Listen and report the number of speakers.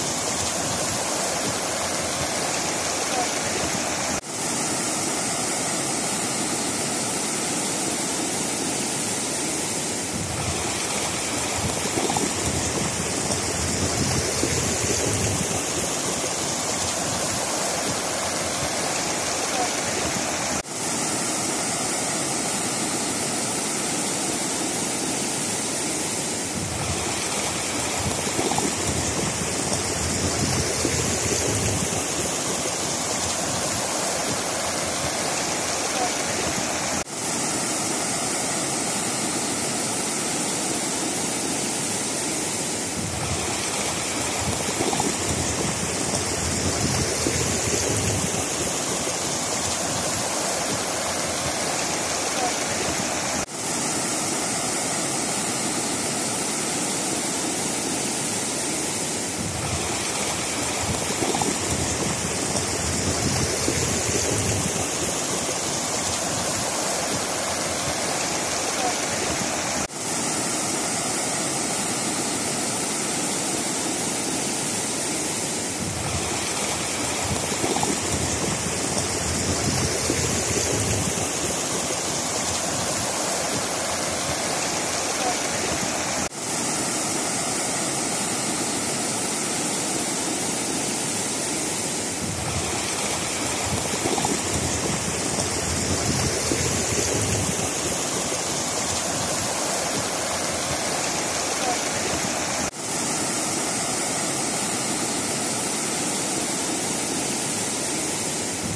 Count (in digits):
0